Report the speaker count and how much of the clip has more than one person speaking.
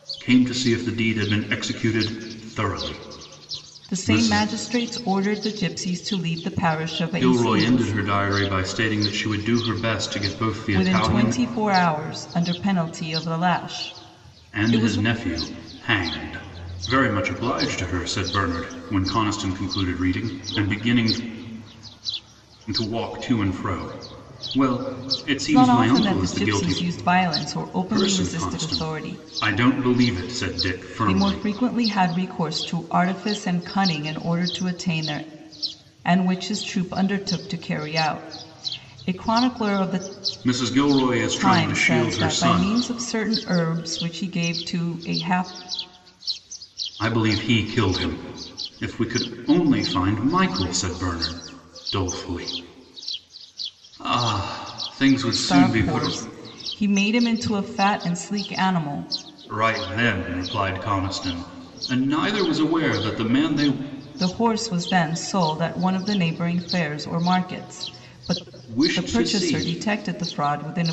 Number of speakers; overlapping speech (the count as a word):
two, about 13%